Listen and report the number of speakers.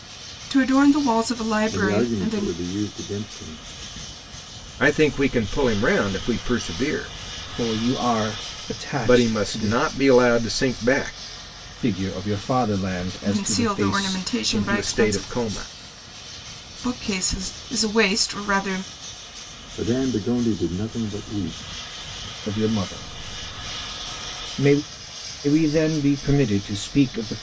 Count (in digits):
4